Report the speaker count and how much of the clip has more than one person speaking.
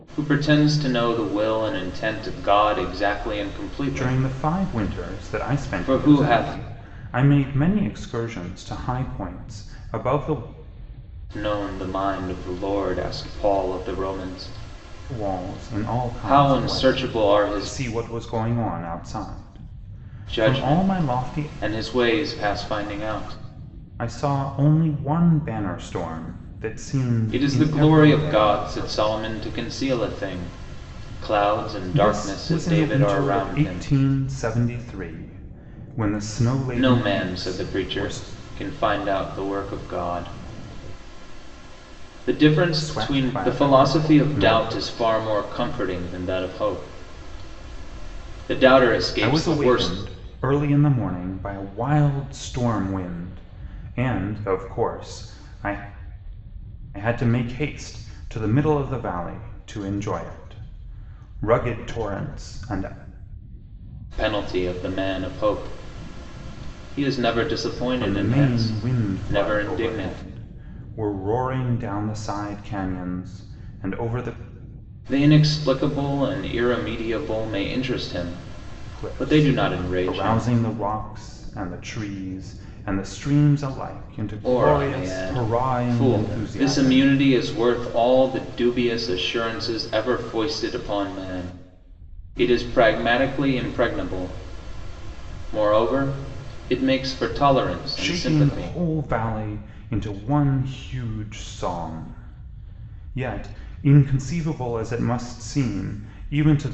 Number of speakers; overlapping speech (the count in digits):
2, about 21%